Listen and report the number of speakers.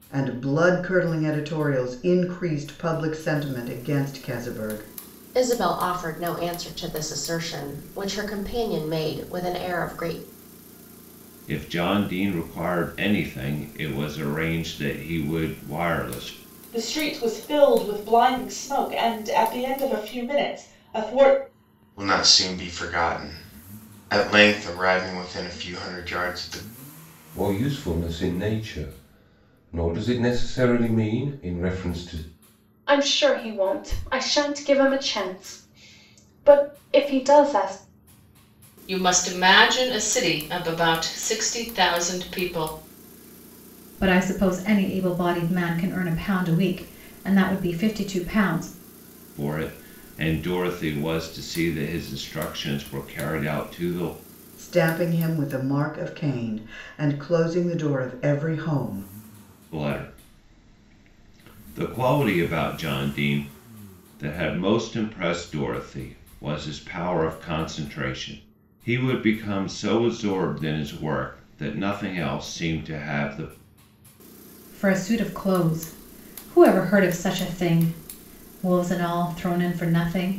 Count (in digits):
9